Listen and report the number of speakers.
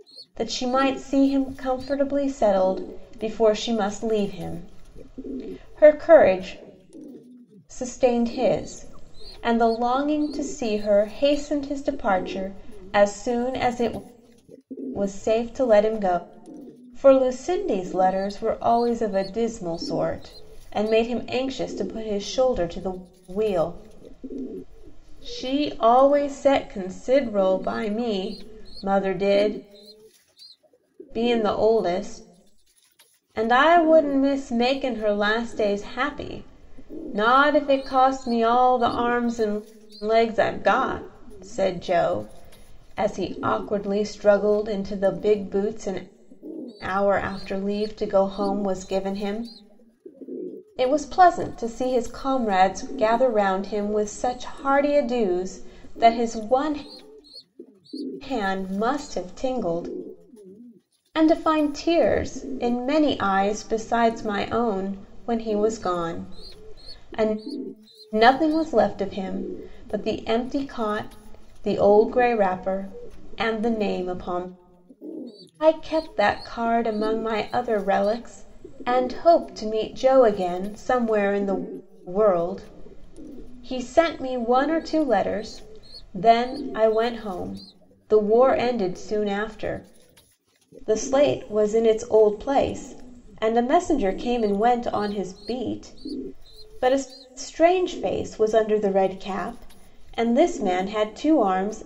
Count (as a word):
one